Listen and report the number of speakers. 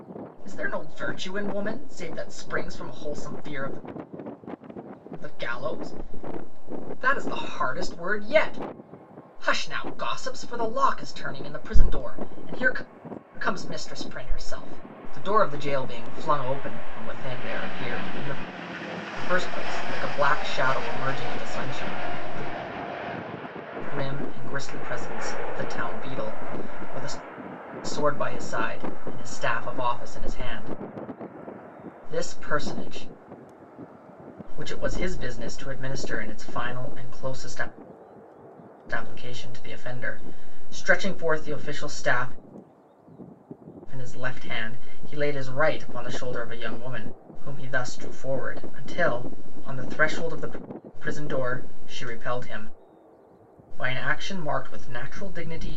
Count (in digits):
1